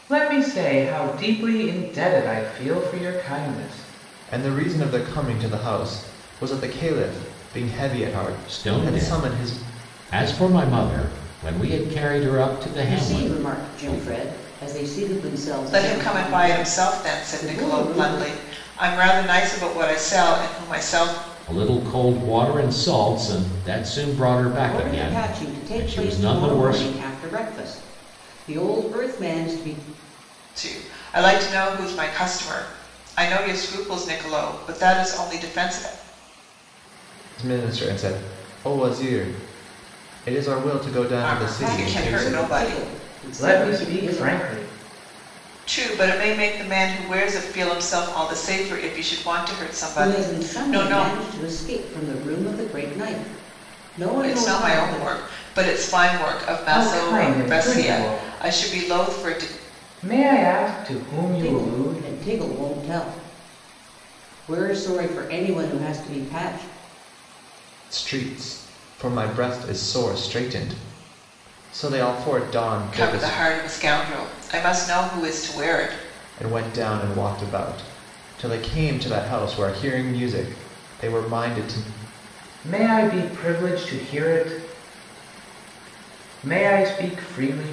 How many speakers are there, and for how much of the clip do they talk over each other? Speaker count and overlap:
5, about 19%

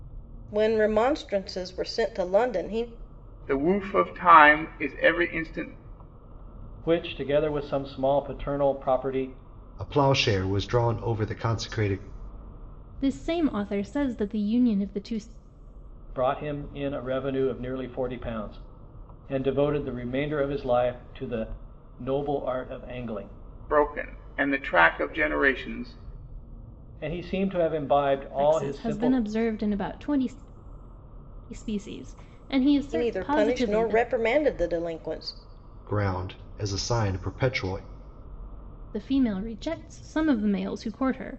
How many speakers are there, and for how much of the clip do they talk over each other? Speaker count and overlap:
5, about 5%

